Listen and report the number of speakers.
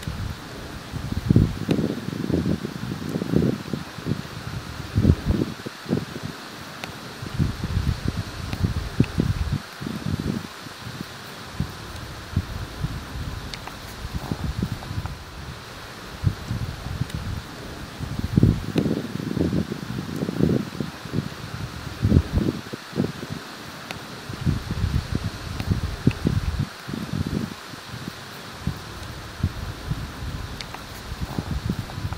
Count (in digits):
0